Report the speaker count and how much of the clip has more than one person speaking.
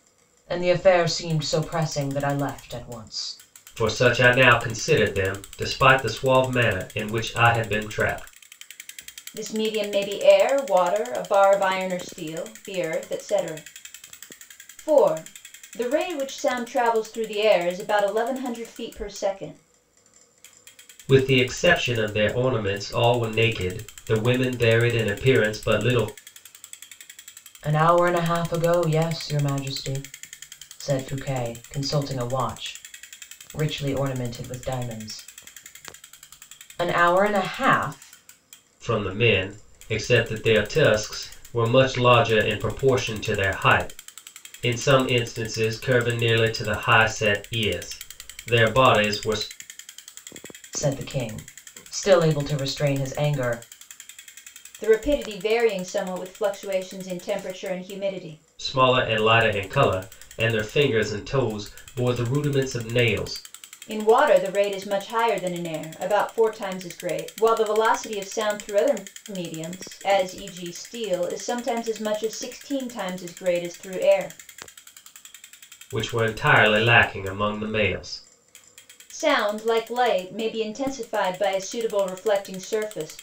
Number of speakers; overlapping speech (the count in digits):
3, no overlap